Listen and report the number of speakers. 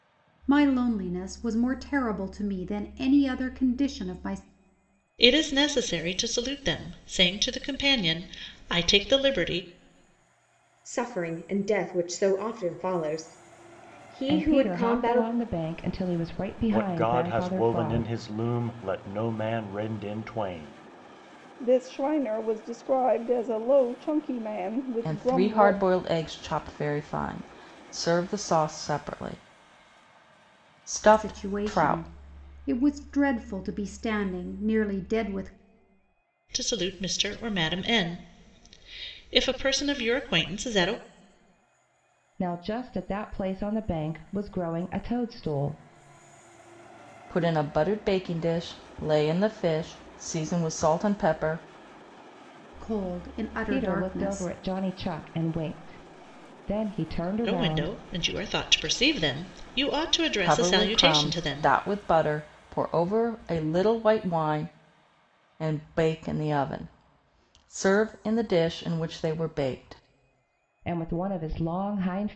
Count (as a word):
seven